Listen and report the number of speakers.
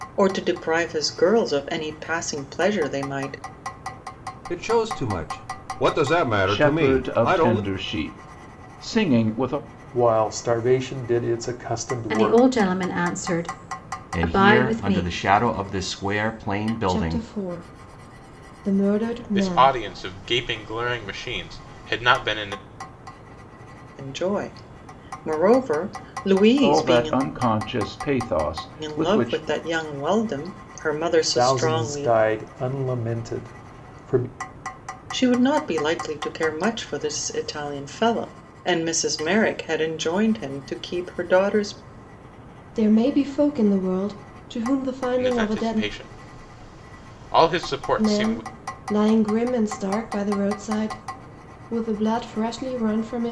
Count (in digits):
8